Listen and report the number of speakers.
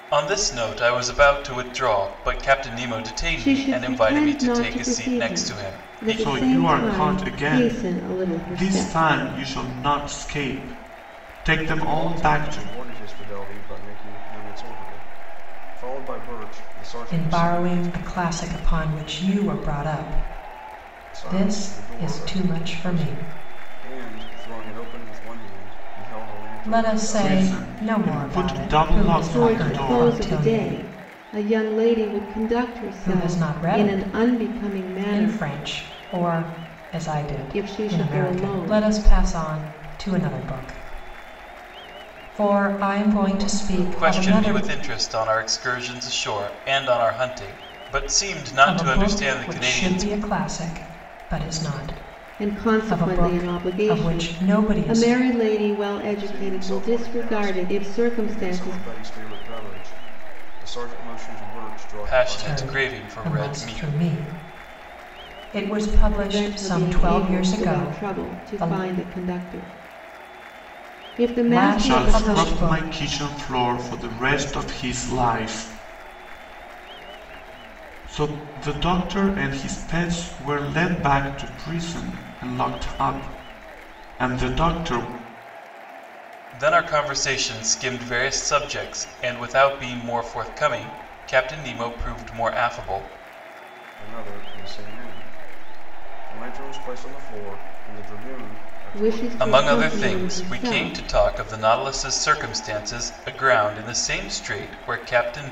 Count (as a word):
five